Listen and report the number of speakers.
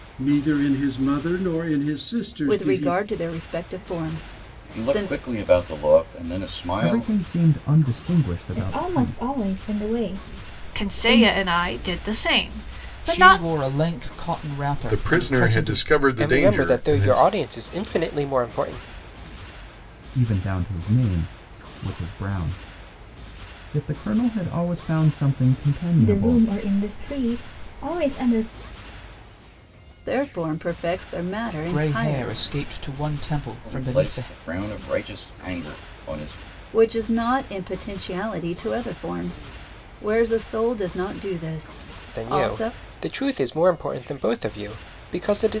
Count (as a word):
nine